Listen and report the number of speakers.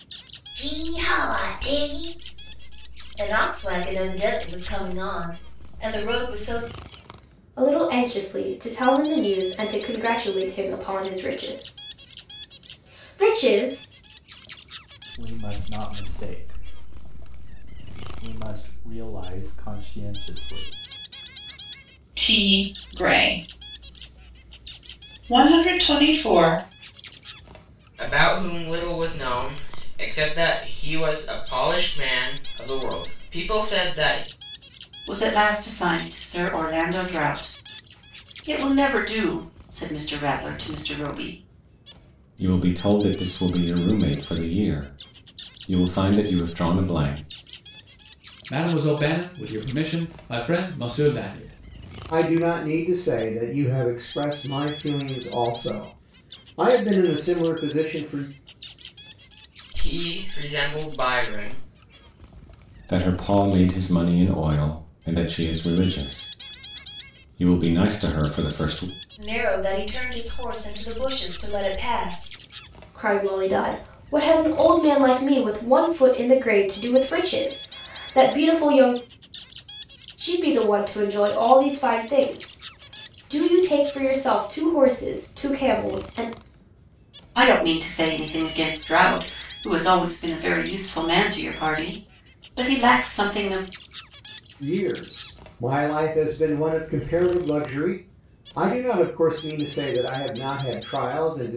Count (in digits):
9